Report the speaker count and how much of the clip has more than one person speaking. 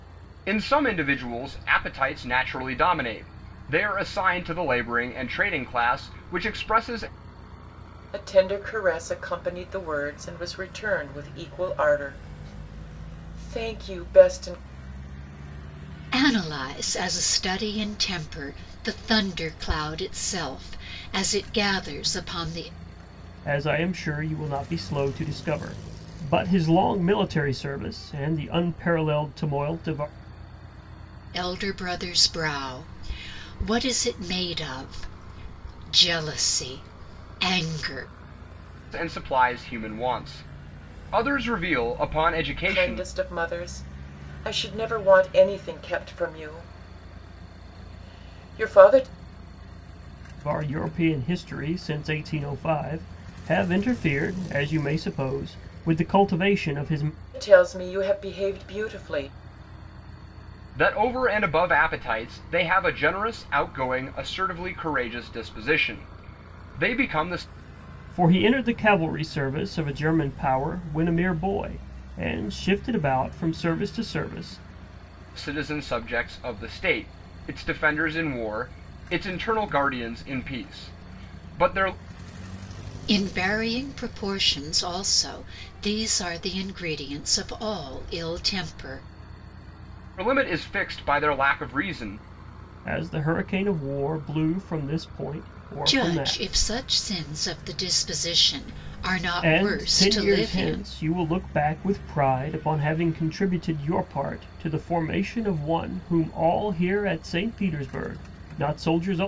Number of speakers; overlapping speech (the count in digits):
4, about 2%